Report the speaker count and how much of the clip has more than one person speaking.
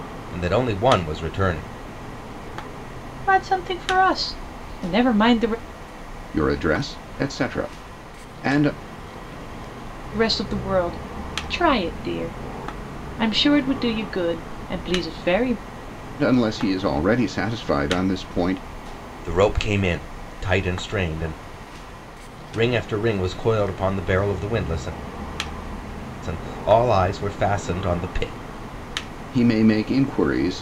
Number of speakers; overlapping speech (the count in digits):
3, no overlap